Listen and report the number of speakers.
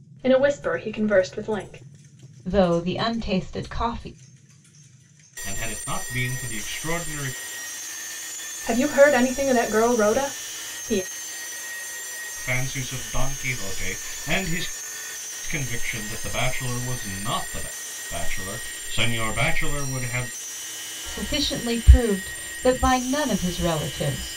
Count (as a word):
three